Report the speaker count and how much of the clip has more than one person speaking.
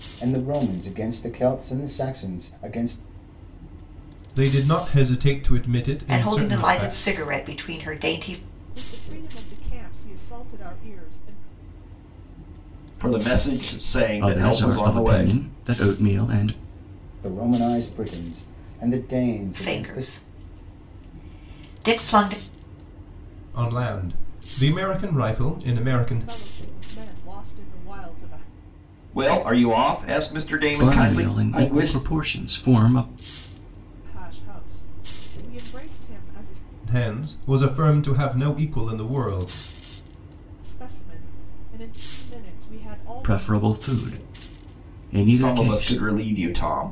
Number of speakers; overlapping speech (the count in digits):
6, about 12%